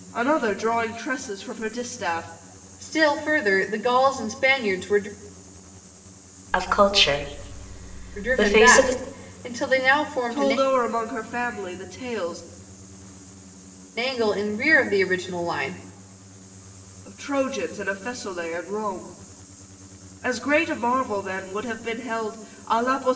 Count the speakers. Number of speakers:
3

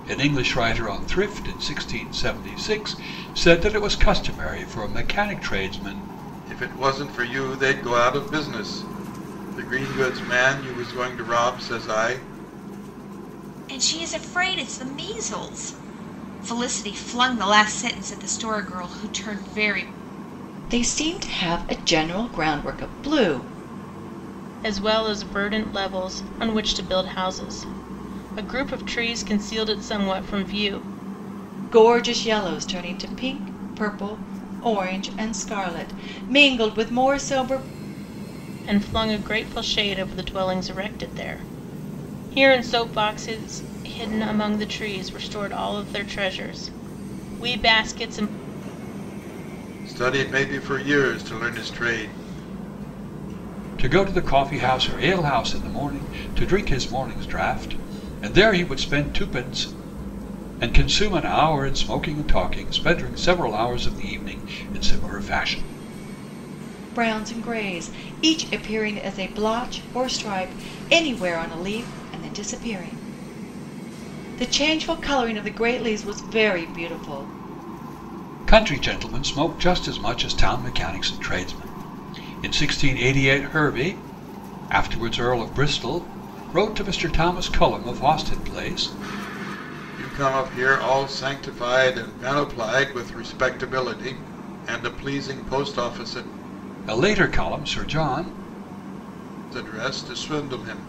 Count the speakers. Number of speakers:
5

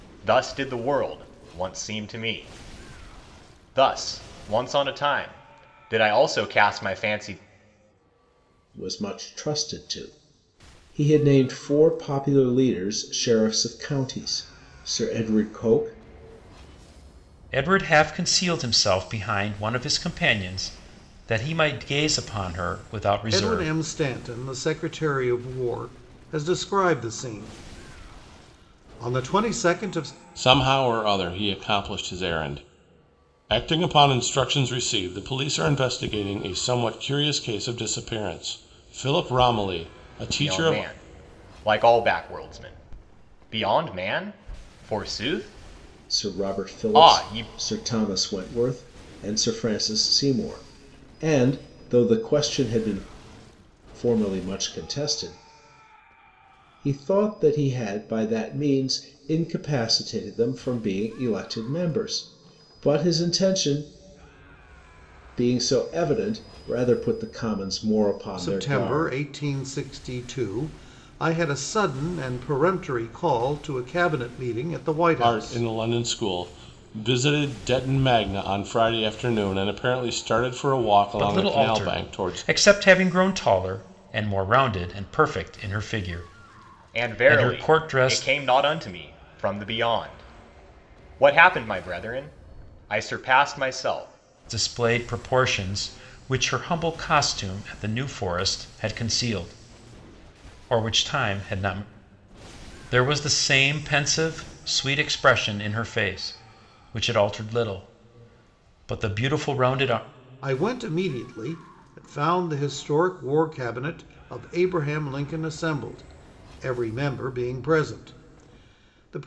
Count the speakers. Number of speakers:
5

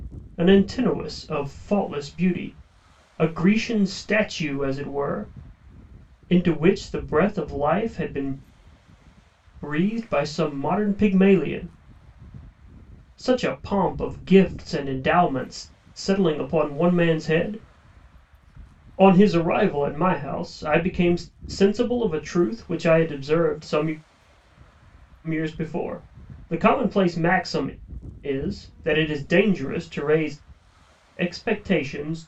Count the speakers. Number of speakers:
1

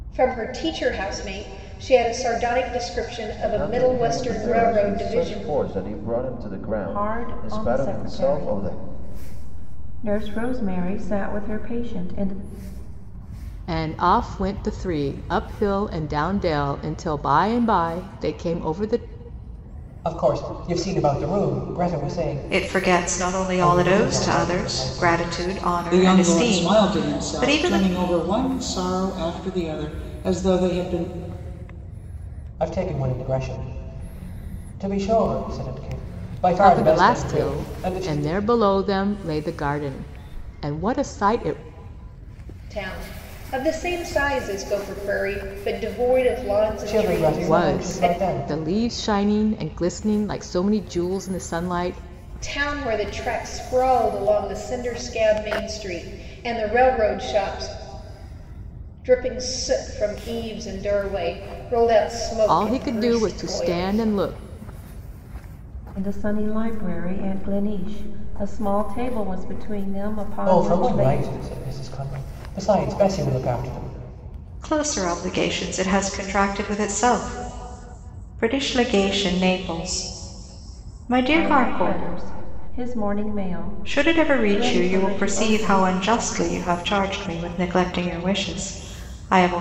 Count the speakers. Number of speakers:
7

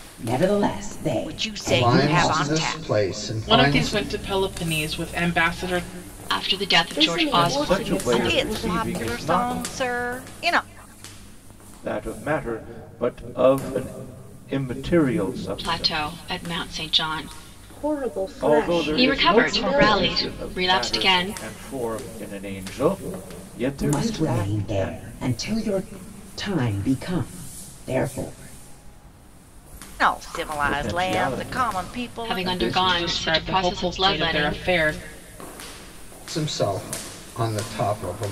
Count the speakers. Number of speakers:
7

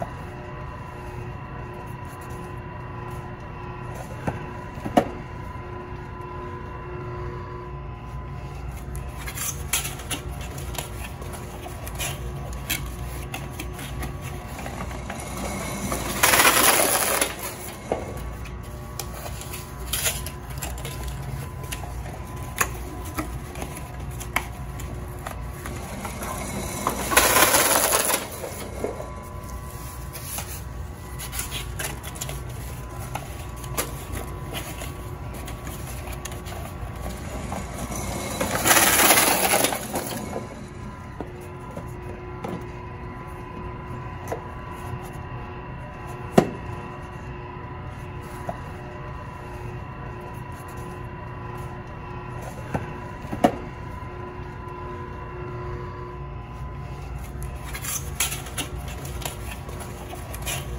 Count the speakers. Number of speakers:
0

